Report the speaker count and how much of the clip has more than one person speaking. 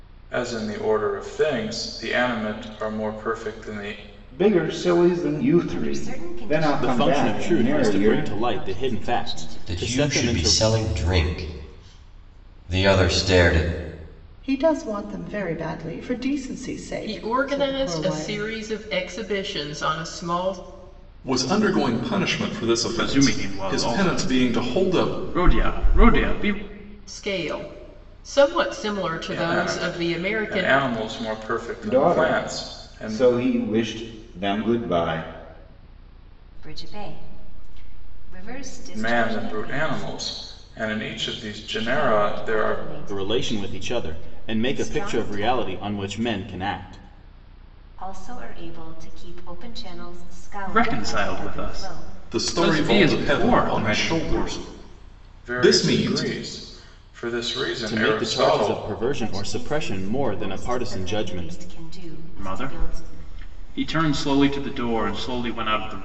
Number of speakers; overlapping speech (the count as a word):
nine, about 38%